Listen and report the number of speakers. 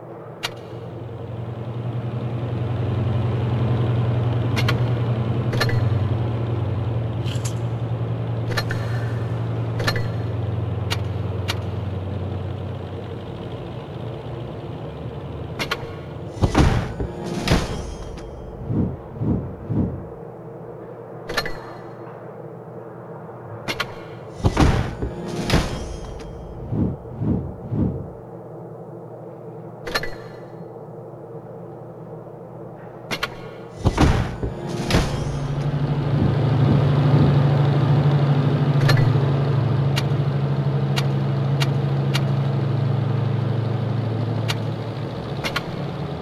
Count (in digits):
0